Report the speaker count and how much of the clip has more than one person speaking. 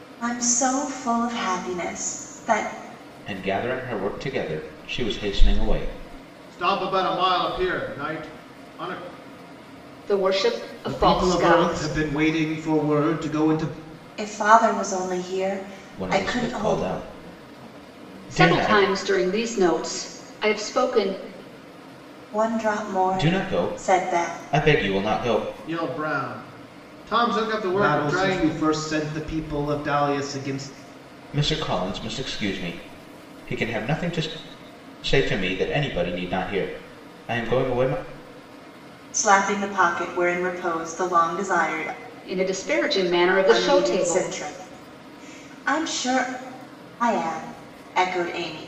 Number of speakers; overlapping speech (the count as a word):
five, about 12%